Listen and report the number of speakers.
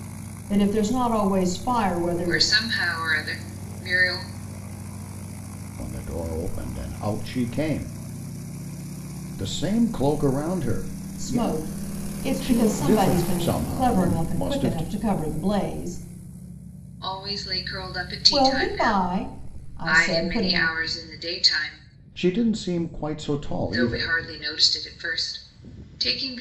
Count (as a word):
three